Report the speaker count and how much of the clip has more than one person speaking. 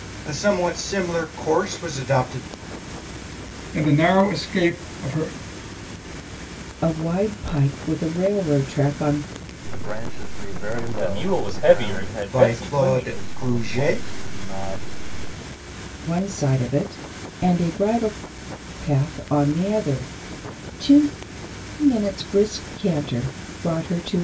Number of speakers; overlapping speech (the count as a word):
five, about 12%